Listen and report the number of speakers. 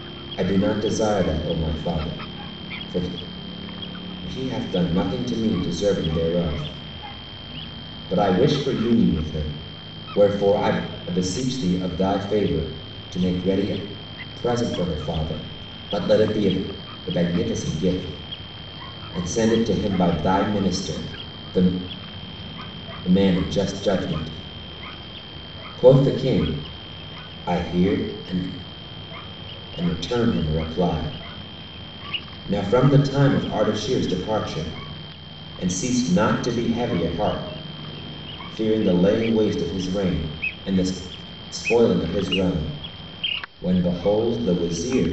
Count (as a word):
one